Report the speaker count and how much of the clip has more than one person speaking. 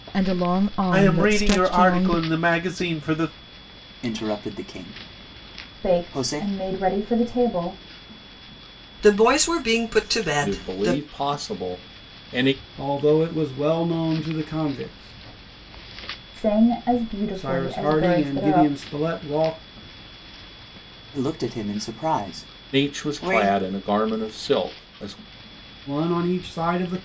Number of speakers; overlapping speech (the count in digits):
7, about 18%